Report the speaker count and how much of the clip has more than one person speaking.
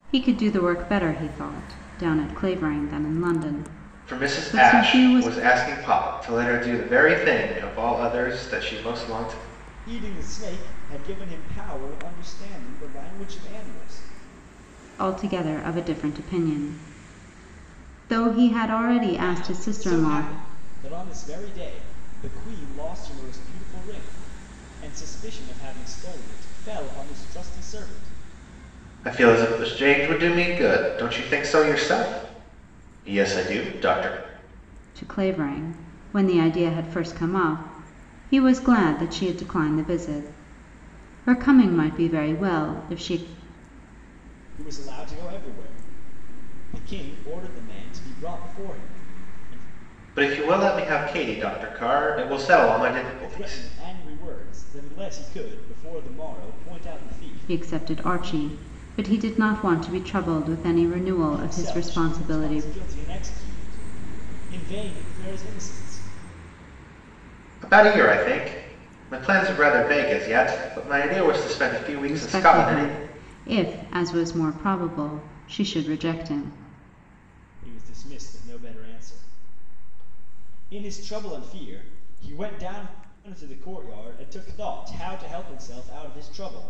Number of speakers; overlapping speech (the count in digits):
3, about 7%